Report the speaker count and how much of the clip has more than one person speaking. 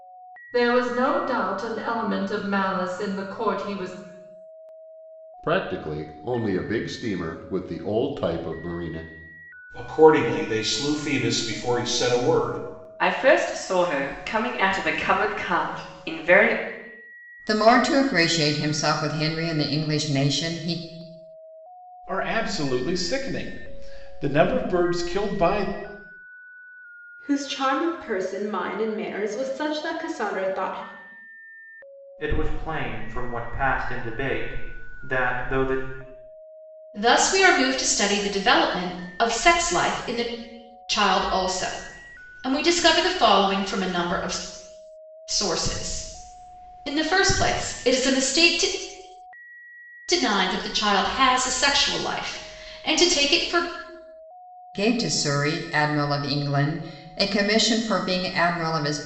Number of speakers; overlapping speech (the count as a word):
nine, no overlap